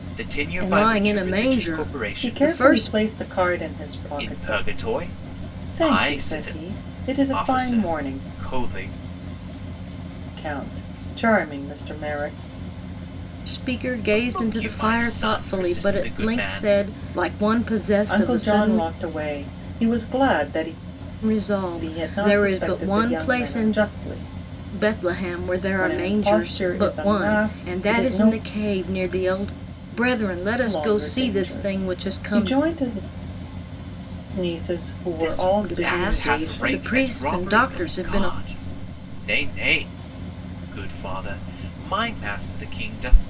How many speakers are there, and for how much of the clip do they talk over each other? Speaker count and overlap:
3, about 42%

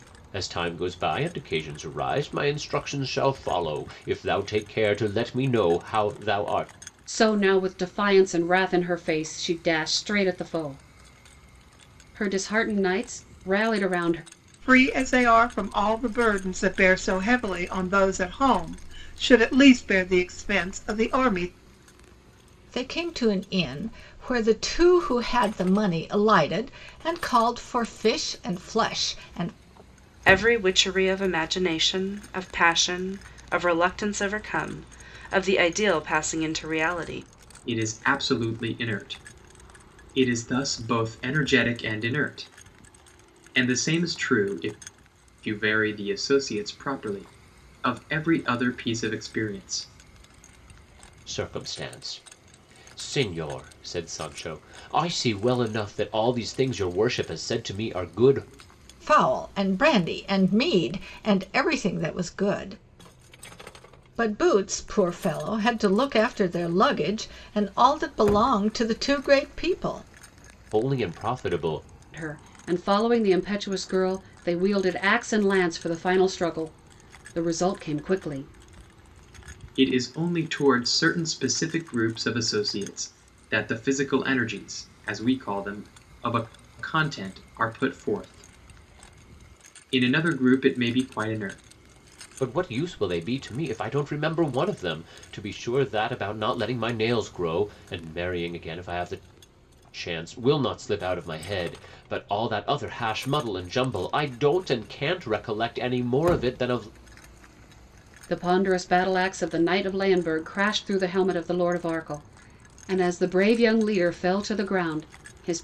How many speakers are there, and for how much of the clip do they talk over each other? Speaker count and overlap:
6, no overlap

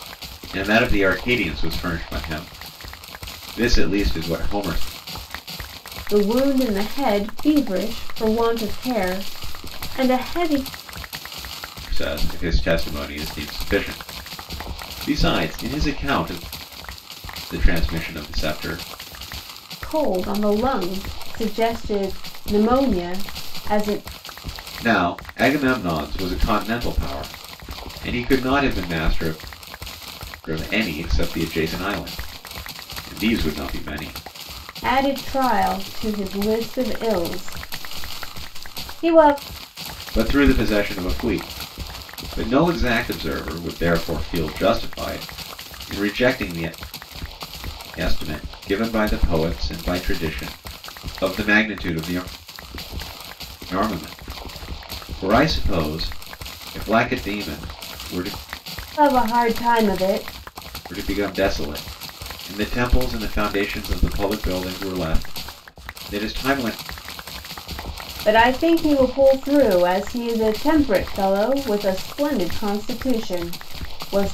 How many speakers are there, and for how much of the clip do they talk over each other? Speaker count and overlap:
2, no overlap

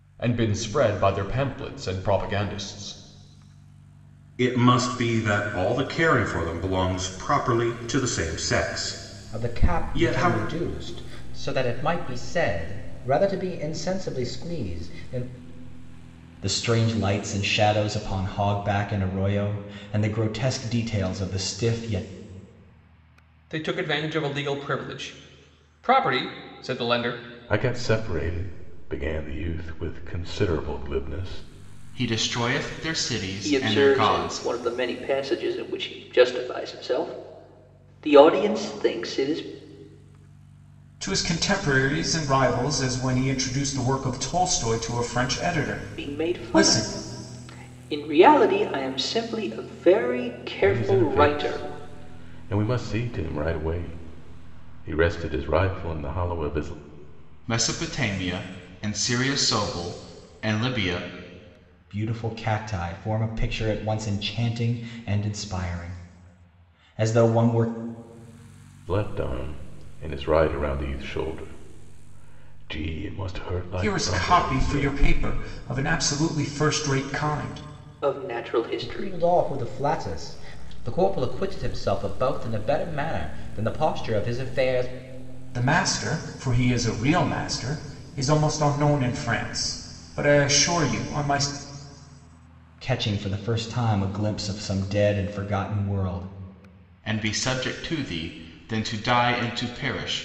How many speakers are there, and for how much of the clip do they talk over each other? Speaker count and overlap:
9, about 6%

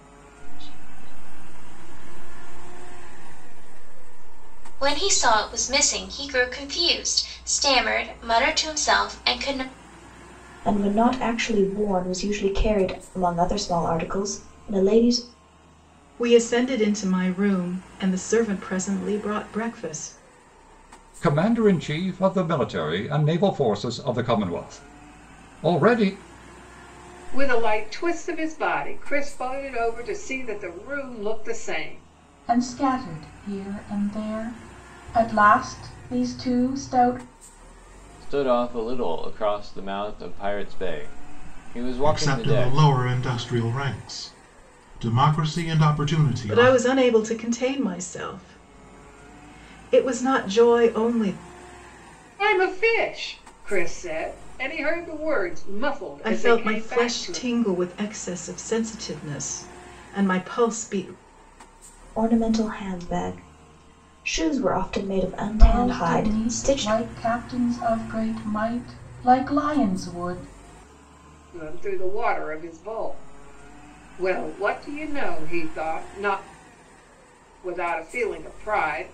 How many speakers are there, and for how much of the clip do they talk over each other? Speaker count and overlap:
9, about 6%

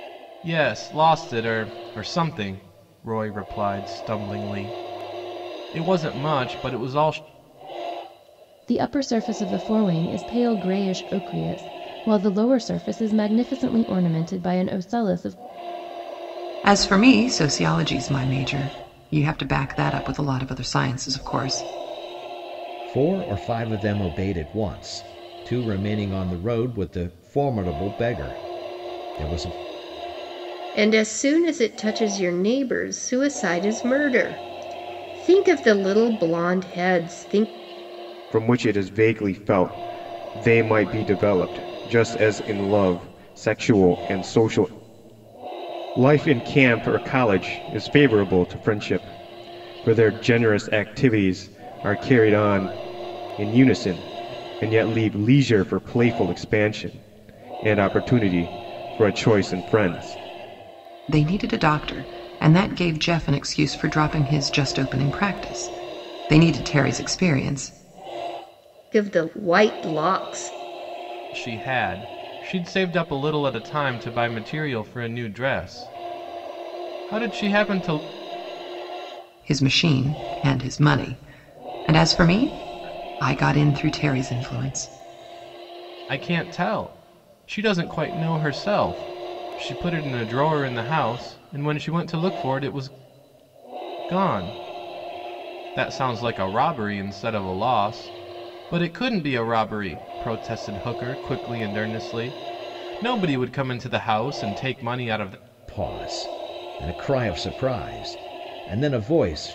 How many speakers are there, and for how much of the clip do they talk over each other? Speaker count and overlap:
6, no overlap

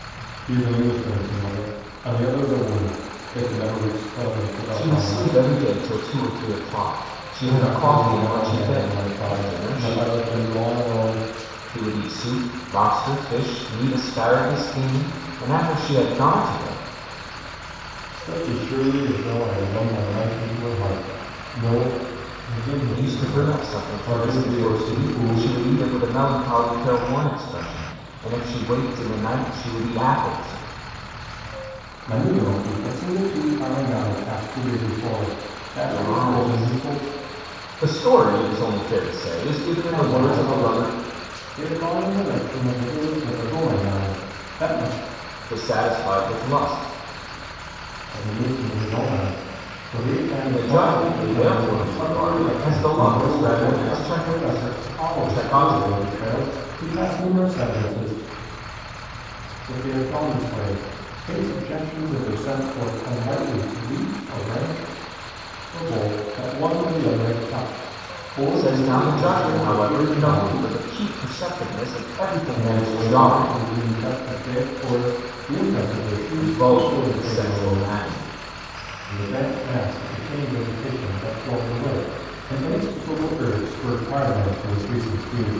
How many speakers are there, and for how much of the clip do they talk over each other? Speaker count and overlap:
2, about 21%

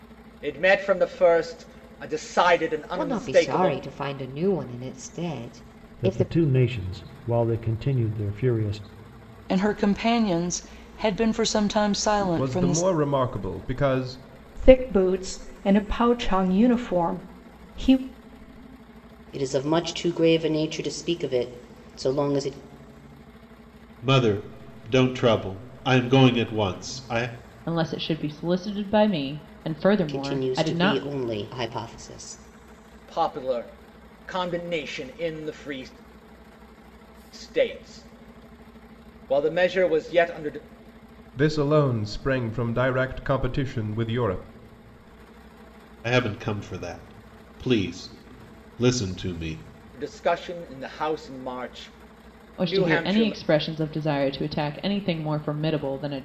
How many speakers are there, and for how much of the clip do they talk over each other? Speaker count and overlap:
9, about 7%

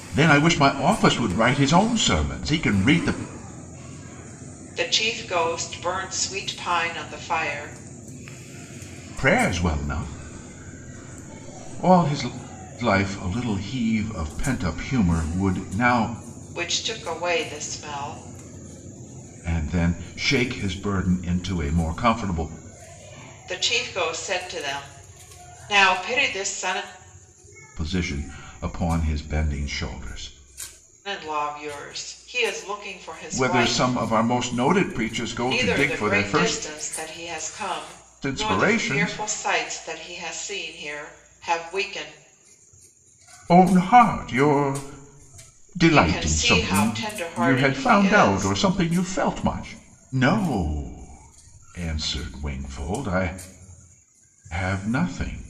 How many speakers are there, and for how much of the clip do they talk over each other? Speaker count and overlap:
2, about 9%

